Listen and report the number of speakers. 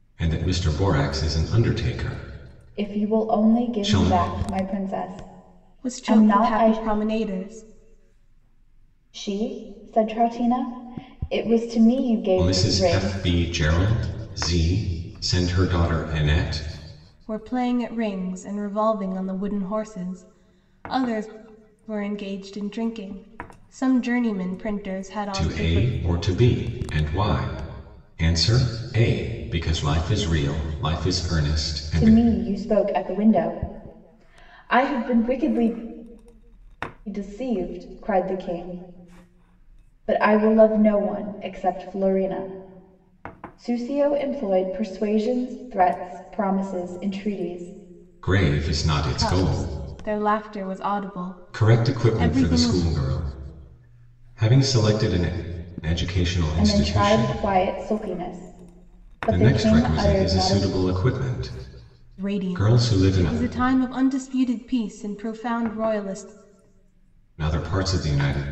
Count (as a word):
three